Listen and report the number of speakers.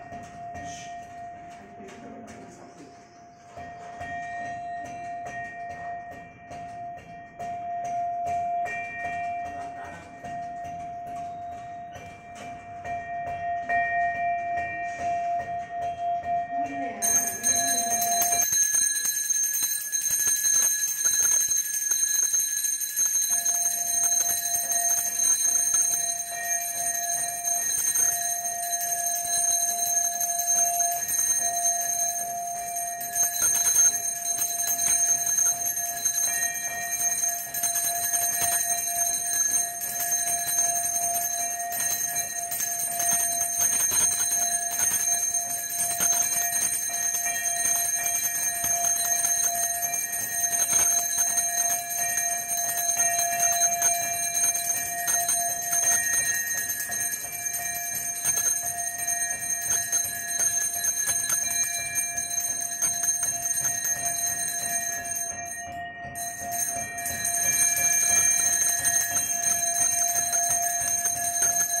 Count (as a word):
zero